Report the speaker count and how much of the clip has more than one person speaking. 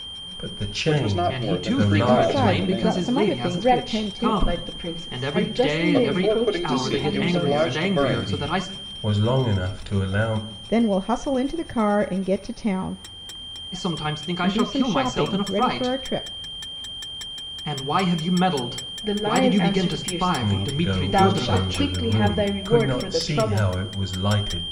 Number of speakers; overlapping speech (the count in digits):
5, about 58%